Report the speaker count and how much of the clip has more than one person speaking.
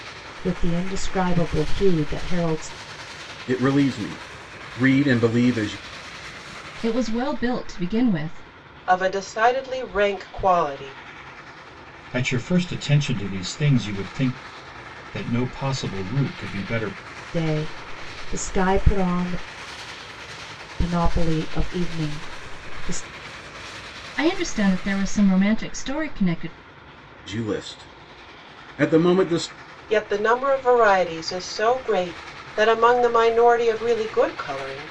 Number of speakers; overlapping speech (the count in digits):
5, no overlap